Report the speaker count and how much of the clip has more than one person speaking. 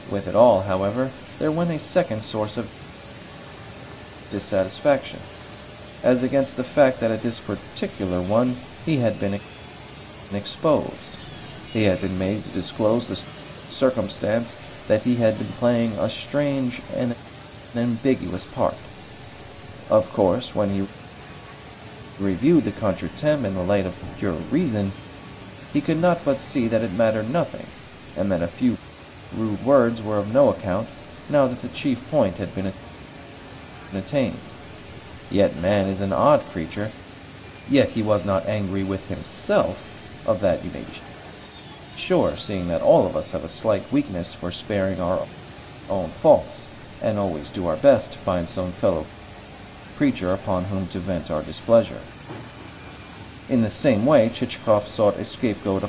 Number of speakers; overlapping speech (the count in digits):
1, no overlap